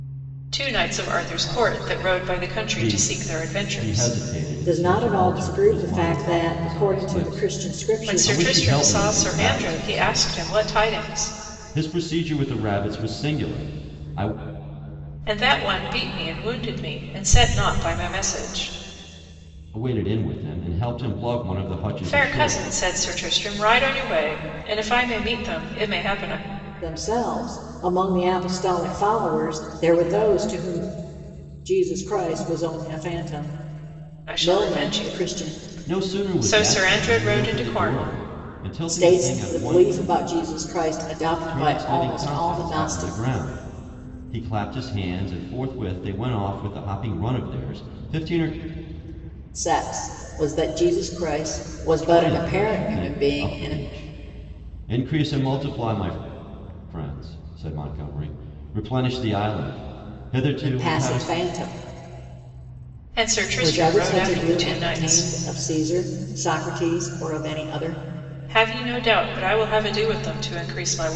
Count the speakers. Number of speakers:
3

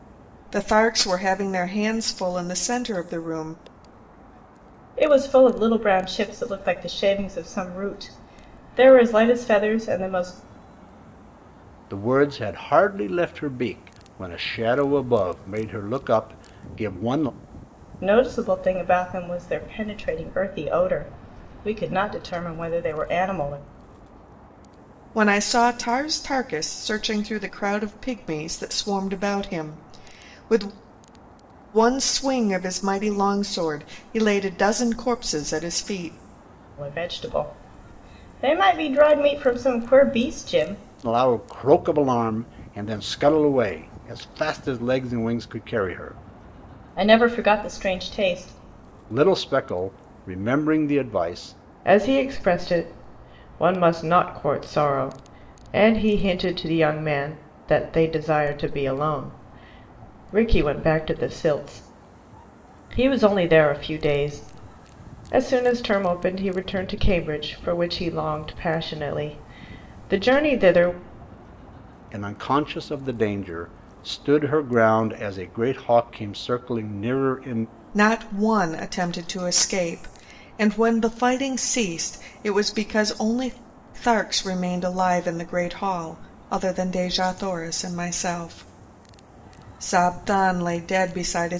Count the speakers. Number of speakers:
3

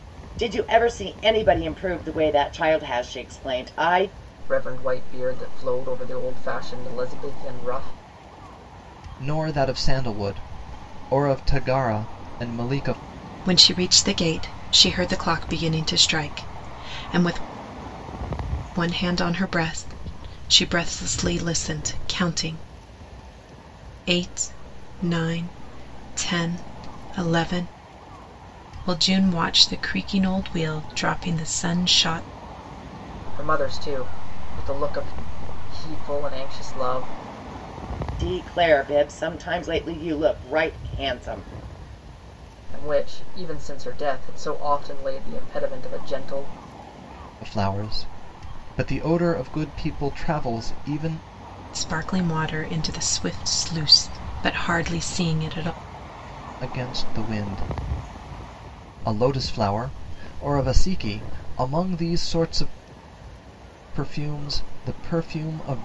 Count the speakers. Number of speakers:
4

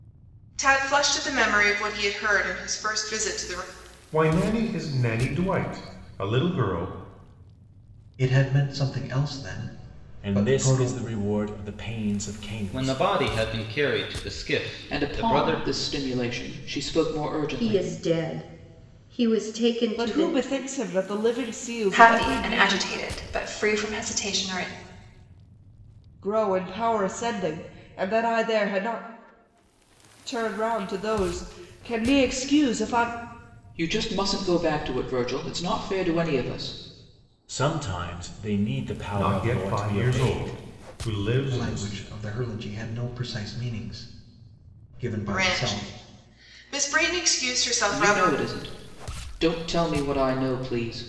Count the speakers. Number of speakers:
9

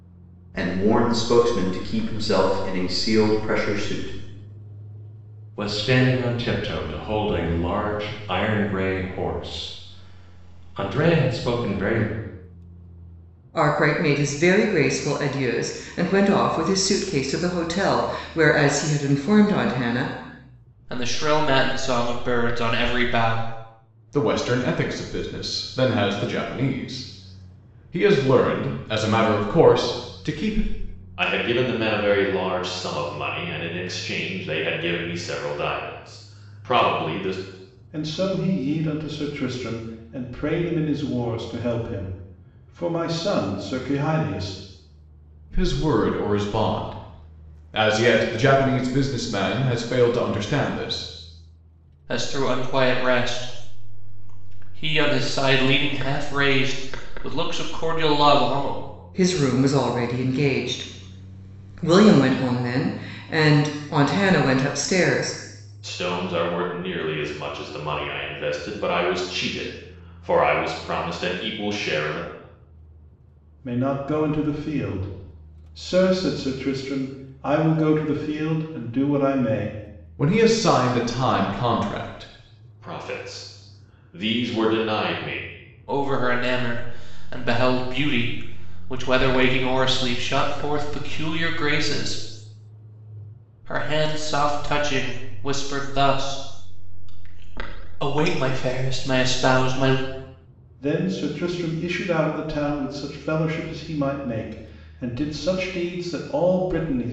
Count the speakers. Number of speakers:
7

